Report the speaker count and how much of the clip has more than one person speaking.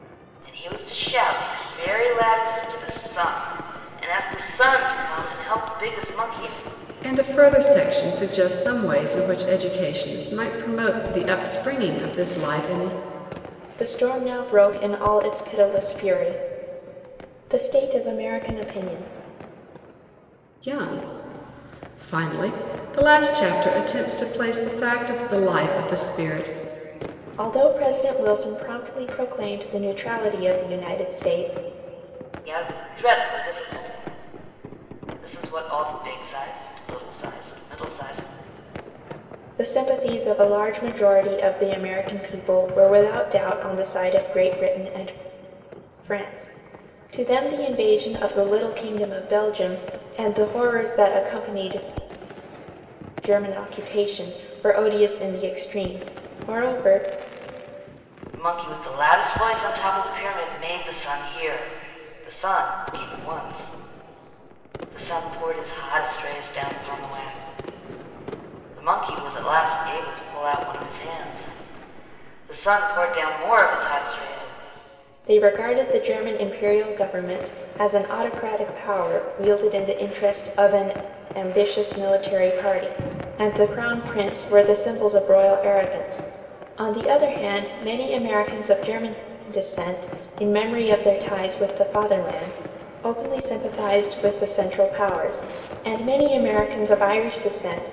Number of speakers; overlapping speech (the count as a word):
three, no overlap